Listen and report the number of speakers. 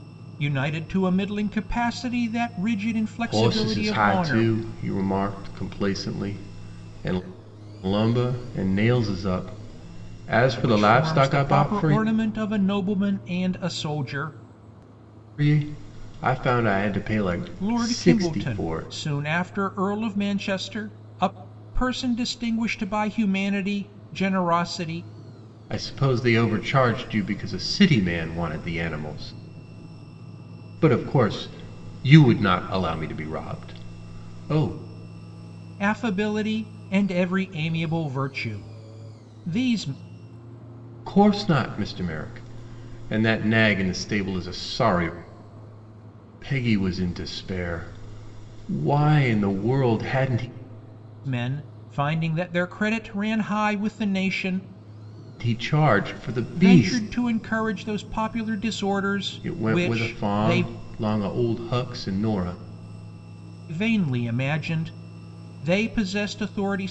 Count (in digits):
2